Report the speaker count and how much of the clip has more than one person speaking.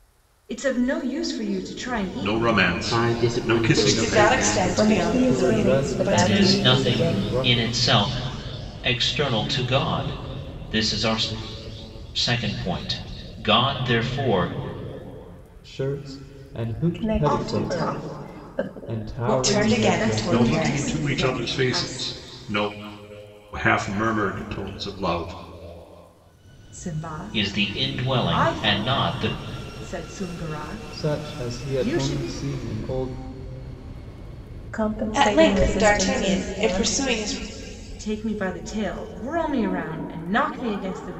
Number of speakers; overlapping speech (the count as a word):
seven, about 38%